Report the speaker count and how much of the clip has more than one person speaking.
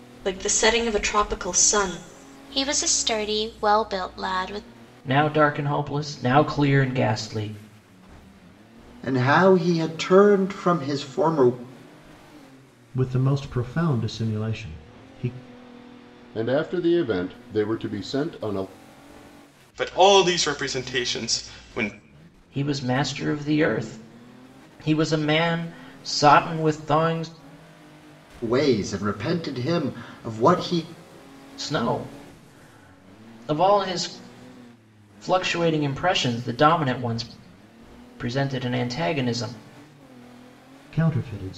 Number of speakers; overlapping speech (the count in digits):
7, no overlap